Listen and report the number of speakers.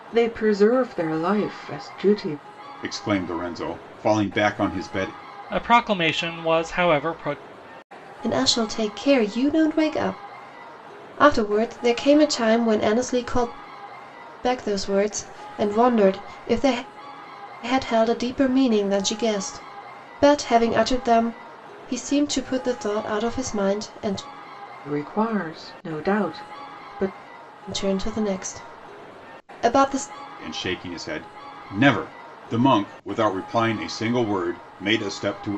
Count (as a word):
four